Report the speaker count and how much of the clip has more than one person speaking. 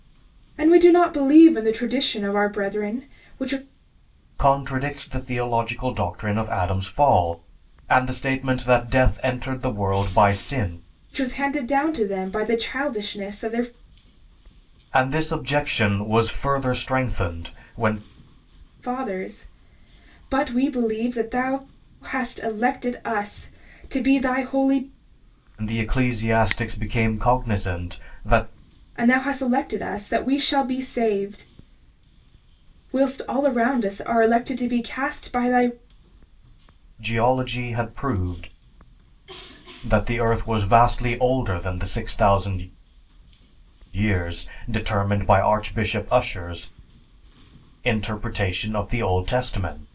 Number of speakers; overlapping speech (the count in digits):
2, no overlap